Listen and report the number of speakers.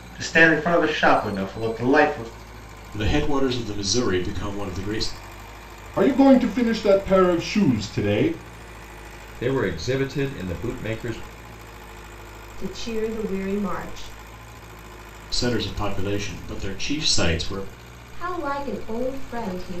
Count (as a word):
five